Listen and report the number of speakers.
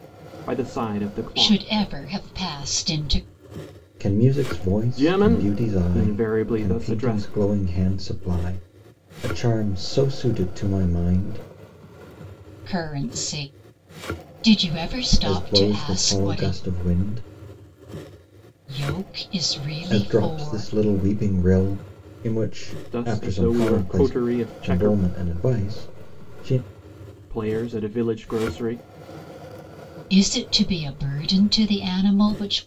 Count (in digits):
3